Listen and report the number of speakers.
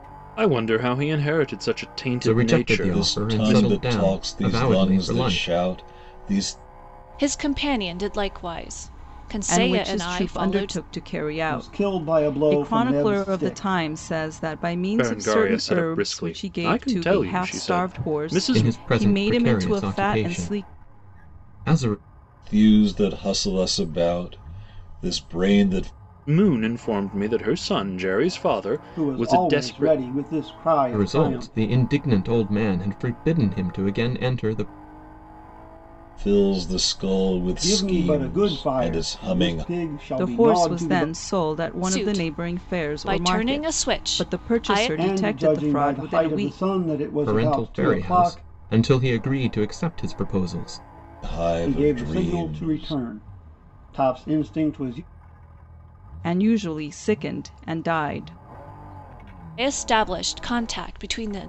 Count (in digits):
6